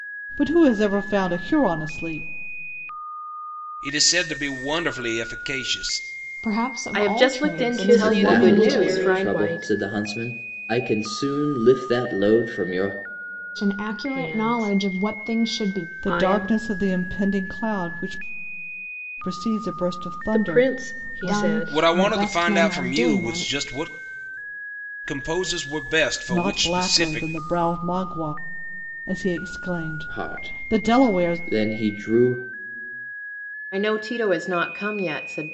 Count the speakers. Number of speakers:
6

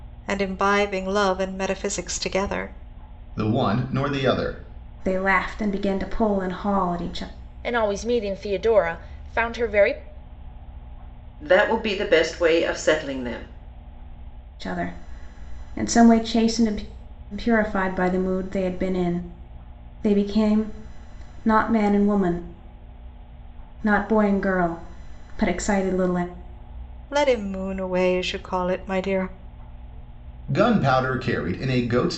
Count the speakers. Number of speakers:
5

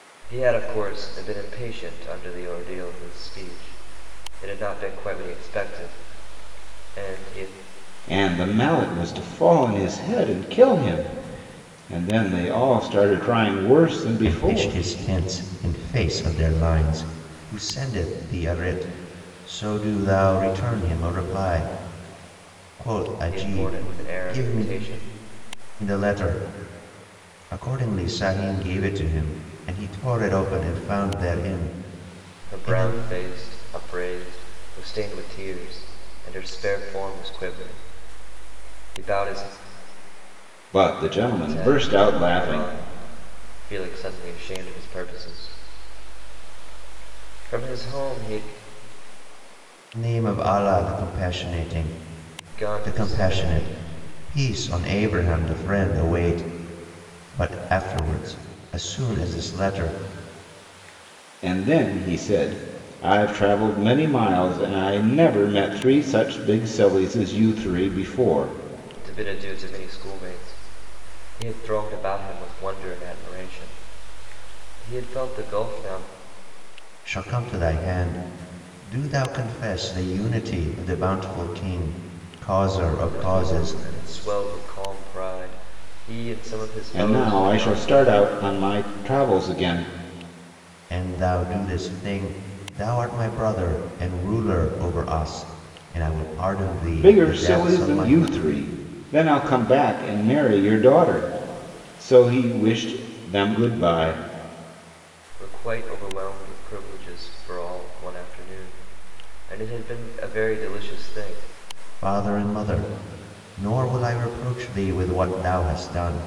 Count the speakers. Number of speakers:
3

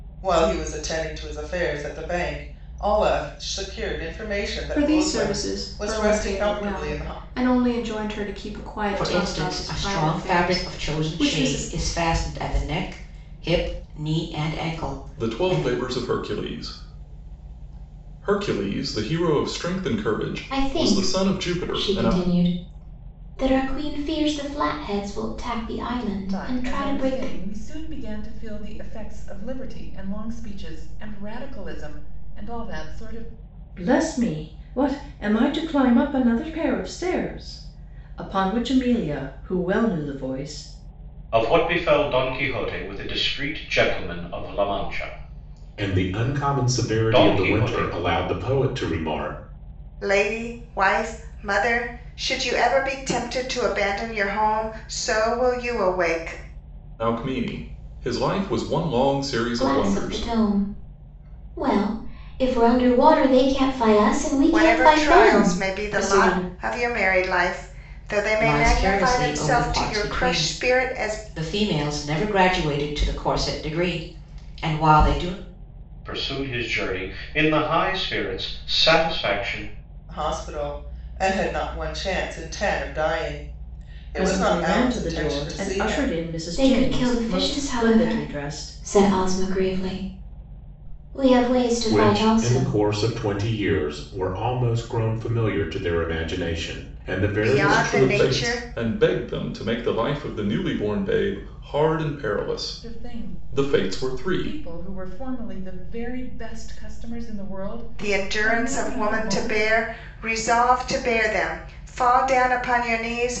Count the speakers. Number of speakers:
10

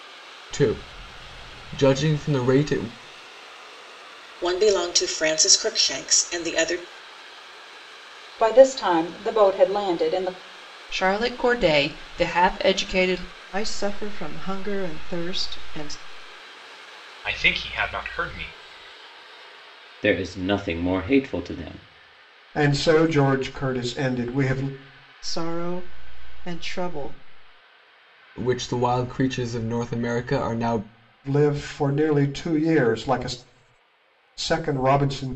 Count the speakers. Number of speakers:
8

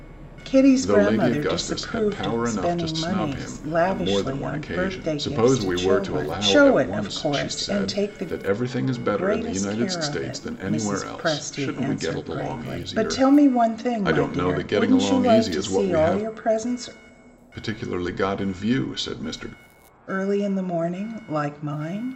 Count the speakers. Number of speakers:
2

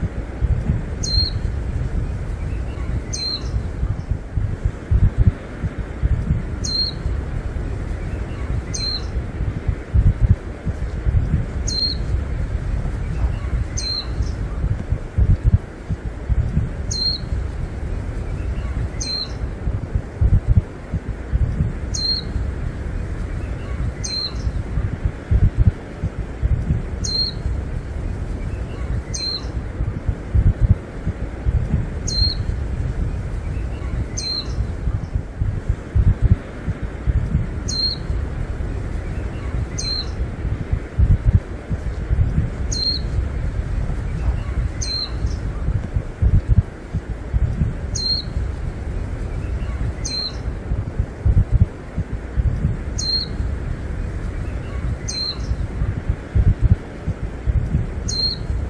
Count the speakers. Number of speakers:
0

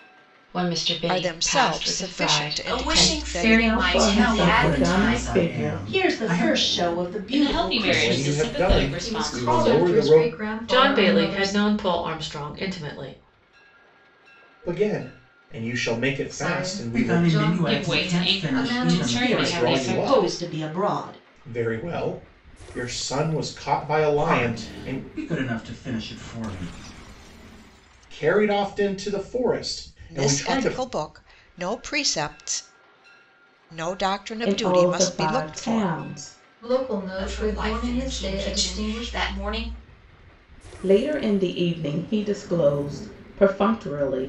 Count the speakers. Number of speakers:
10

